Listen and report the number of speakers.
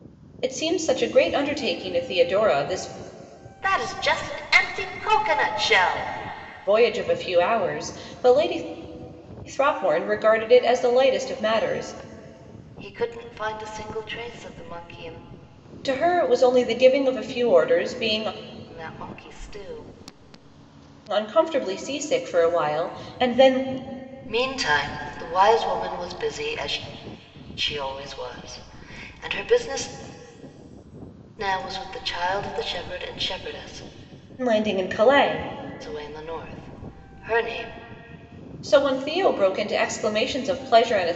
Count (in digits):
2